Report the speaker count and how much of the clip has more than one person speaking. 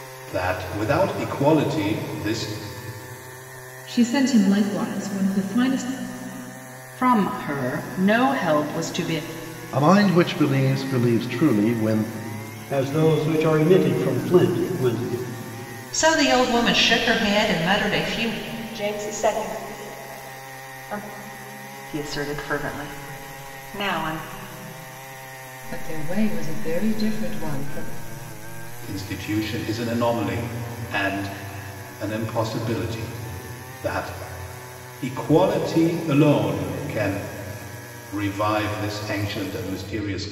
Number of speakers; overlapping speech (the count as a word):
nine, no overlap